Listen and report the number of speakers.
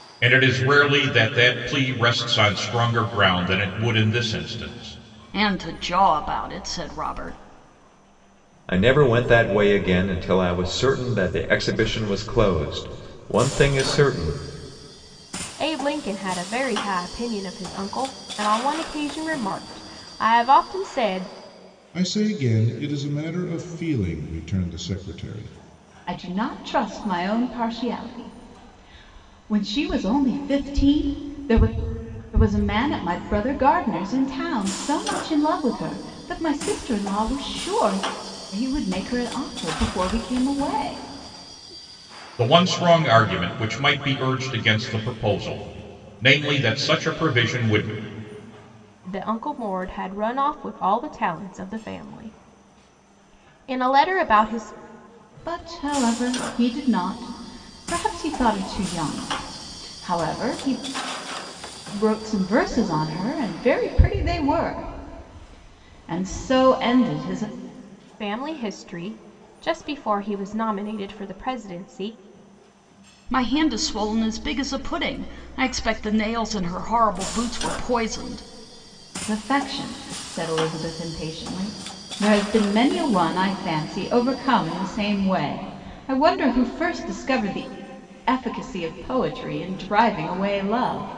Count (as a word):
six